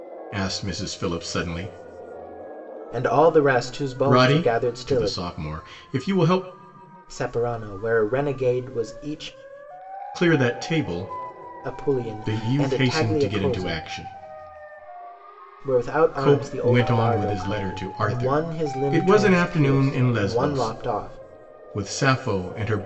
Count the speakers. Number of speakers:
2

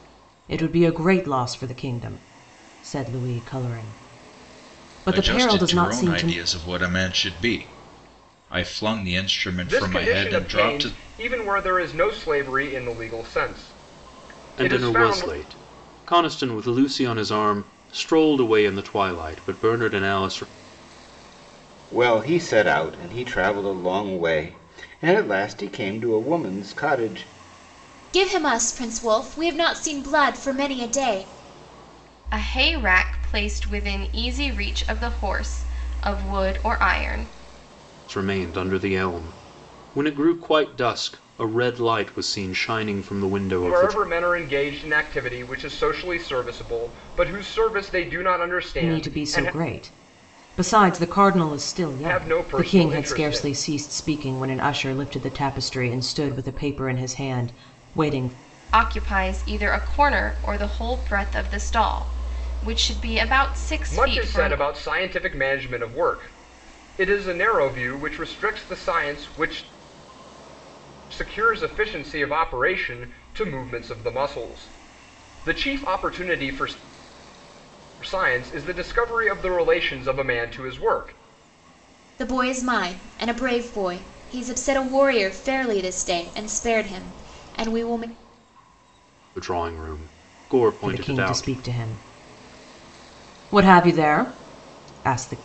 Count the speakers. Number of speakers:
7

